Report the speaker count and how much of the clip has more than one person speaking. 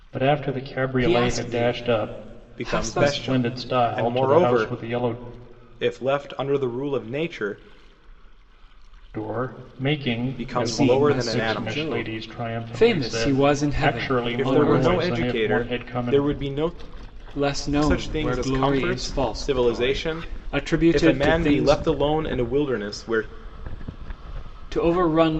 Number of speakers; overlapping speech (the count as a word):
three, about 47%